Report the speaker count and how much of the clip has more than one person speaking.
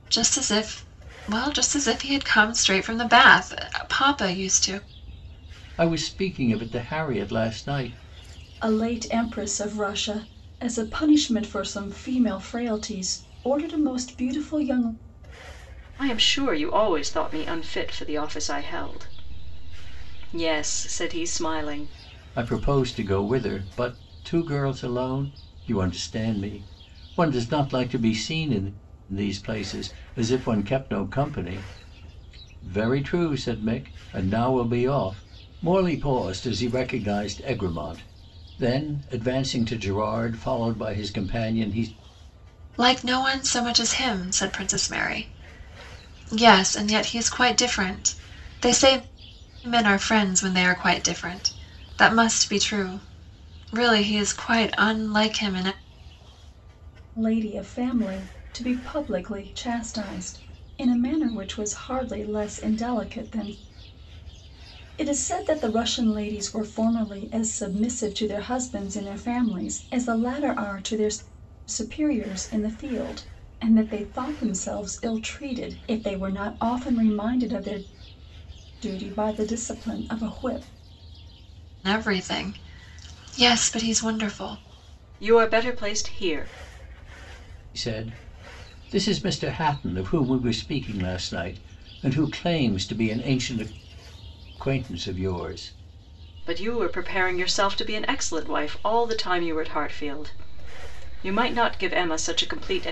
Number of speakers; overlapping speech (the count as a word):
four, no overlap